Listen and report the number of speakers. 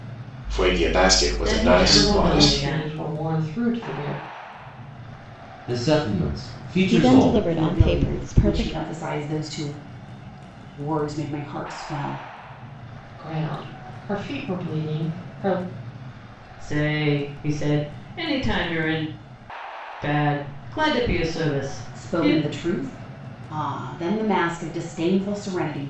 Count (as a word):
six